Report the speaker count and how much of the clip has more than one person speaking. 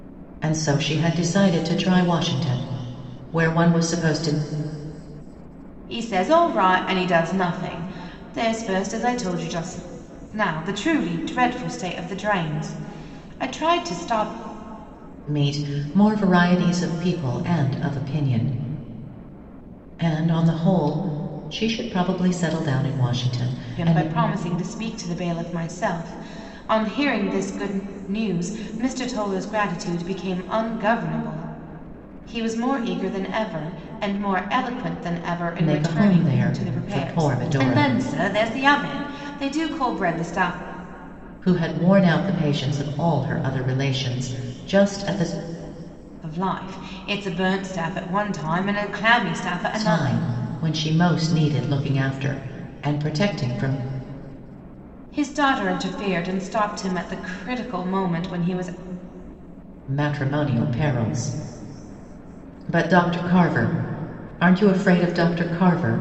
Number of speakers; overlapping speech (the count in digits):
2, about 5%